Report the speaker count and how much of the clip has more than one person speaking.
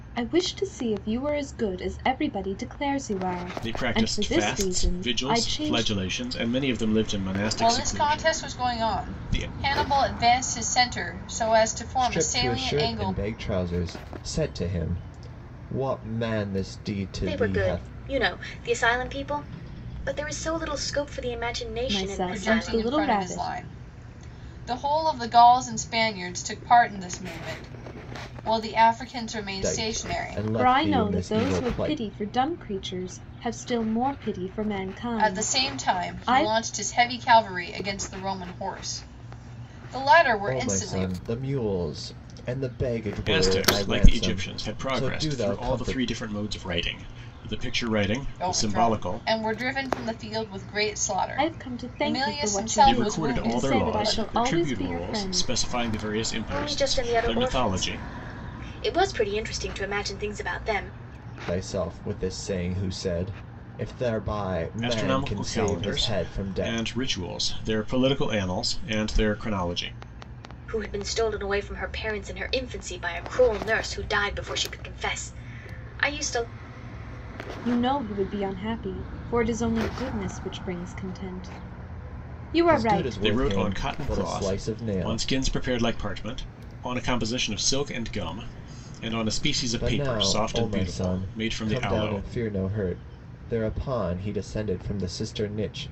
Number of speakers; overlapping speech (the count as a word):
five, about 31%